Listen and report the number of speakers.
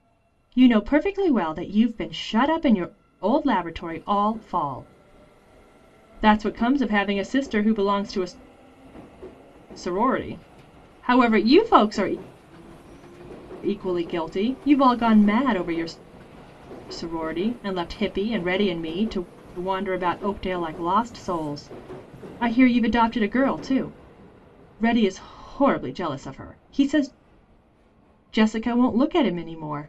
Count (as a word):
one